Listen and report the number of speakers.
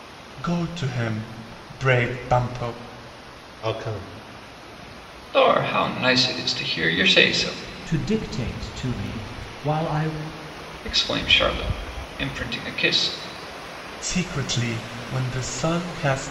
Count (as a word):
four